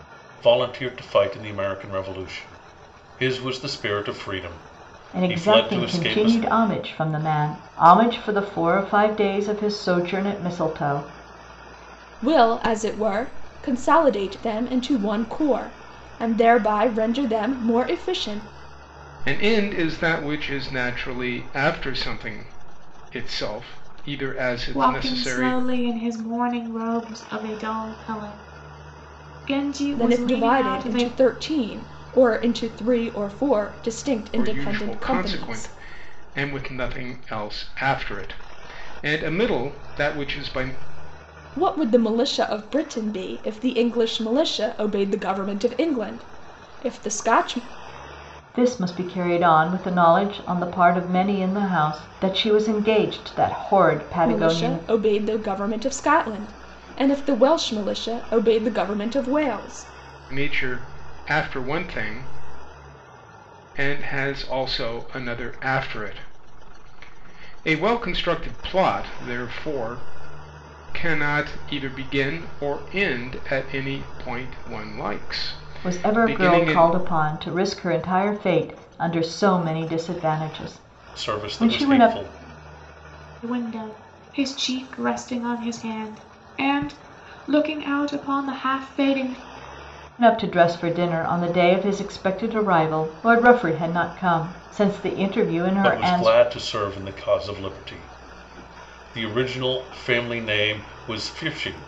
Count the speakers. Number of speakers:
five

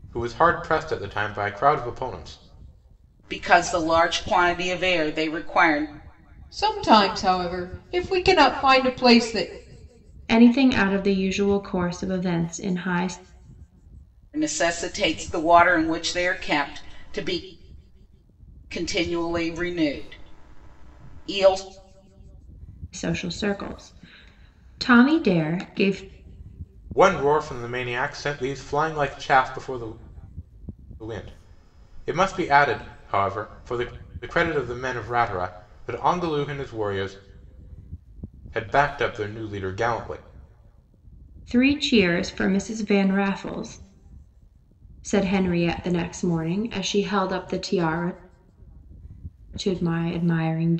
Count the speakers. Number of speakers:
four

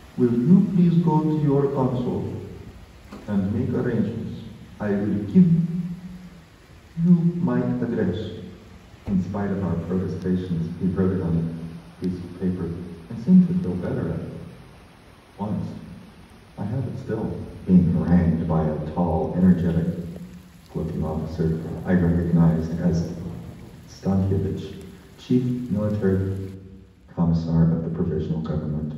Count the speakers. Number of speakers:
one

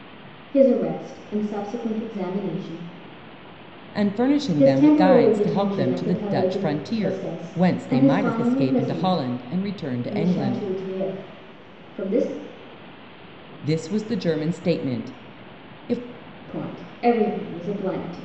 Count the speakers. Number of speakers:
two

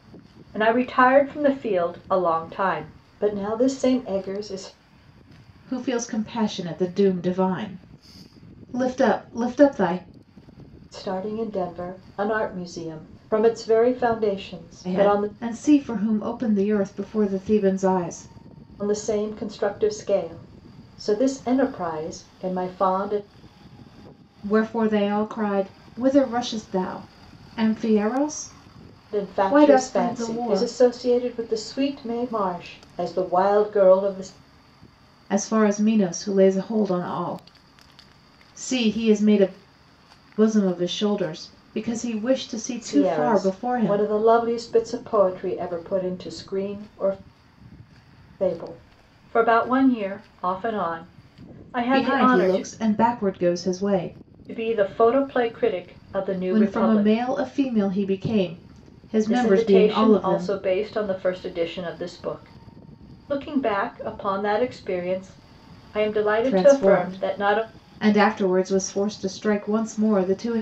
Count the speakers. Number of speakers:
two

